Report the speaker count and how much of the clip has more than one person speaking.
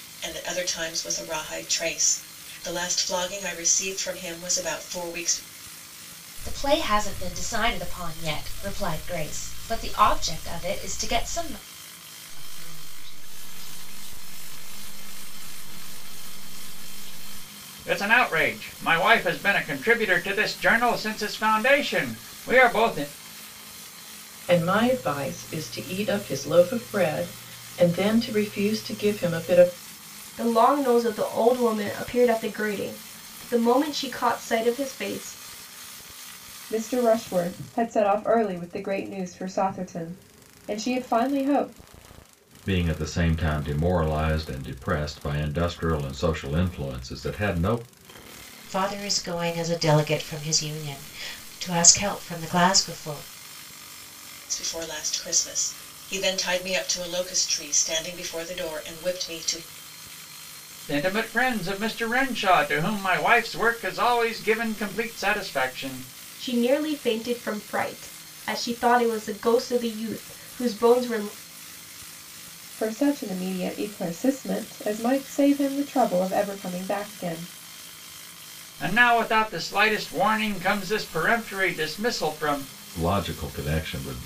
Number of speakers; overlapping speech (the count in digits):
9, no overlap